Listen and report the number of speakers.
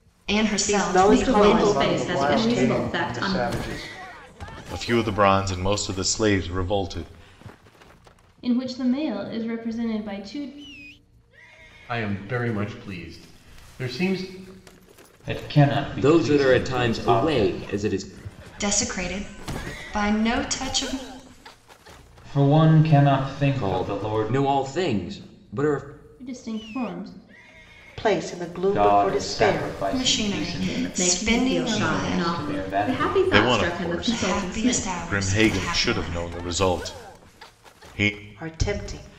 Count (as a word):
nine